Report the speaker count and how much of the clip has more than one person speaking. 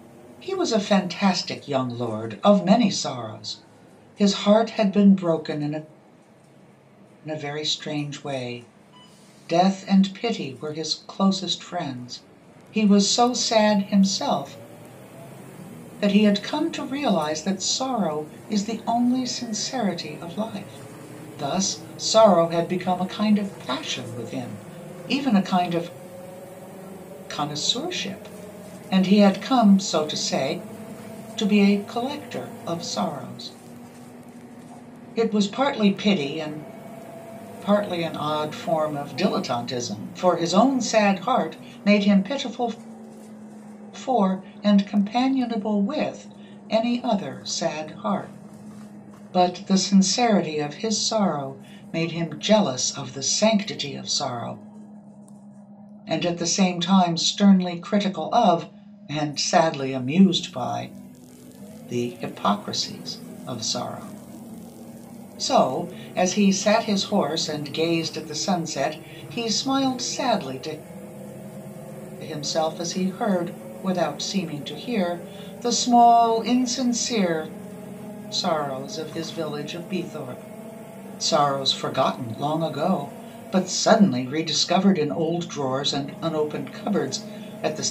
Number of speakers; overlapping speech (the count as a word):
one, no overlap